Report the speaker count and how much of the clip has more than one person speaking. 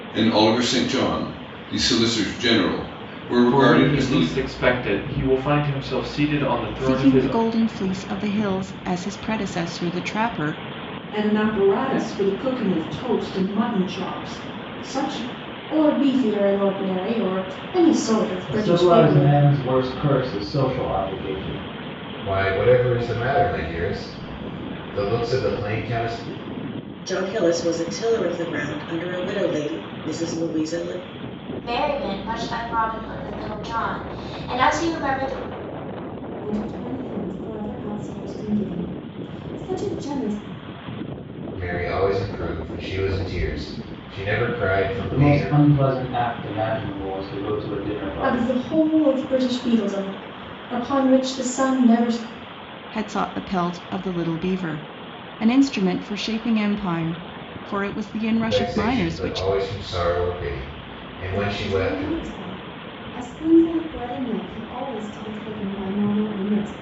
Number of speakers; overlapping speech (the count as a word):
ten, about 8%